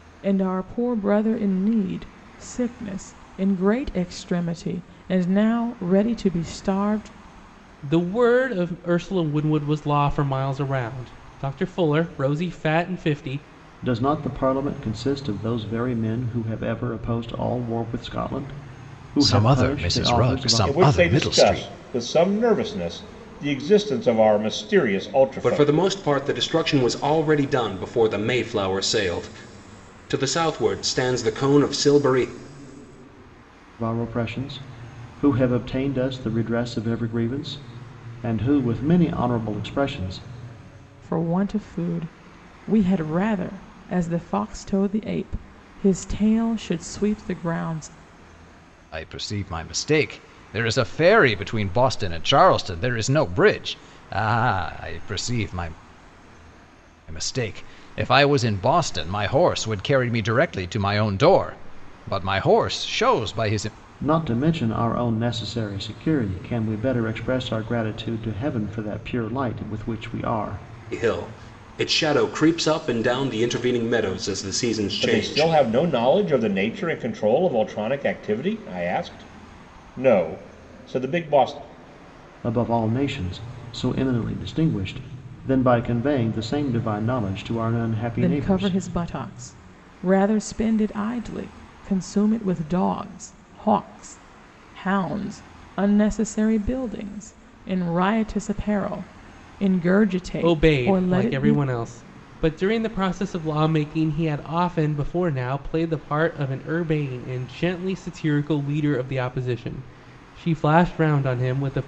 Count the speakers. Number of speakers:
six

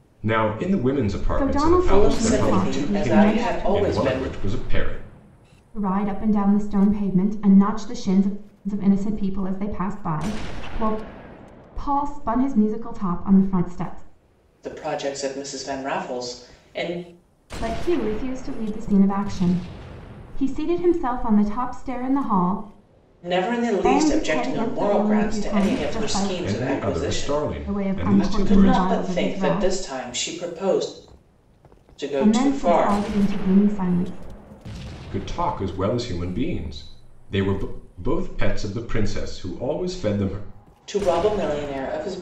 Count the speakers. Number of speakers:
three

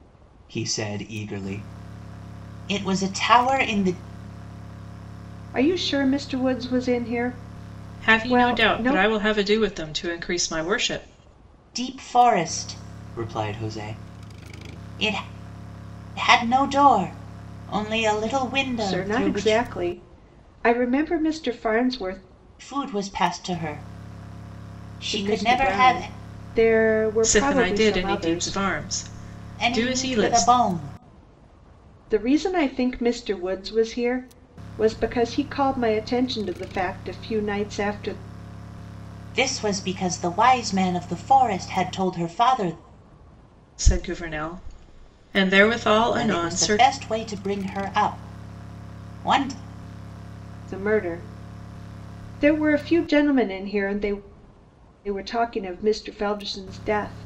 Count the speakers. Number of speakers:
three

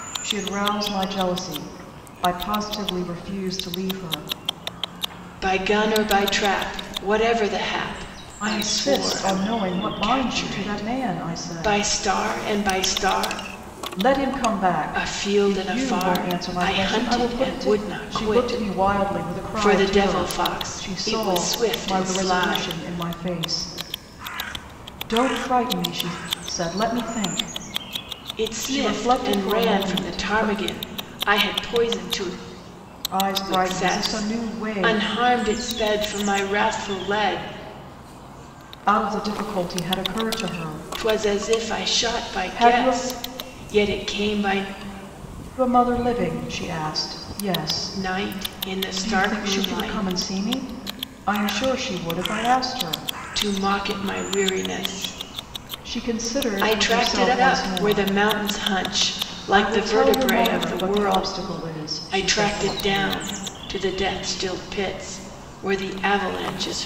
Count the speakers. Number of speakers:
two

